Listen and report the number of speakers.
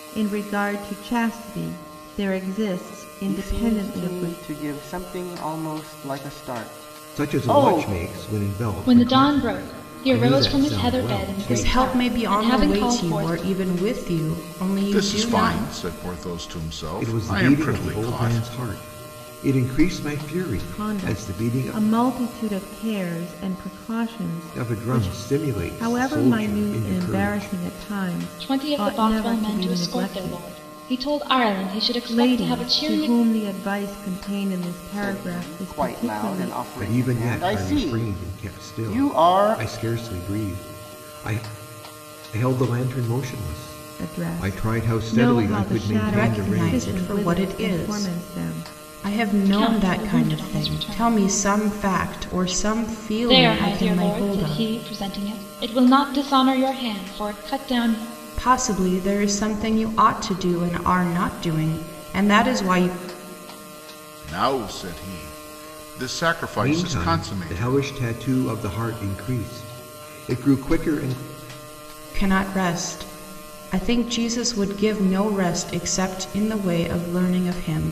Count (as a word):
six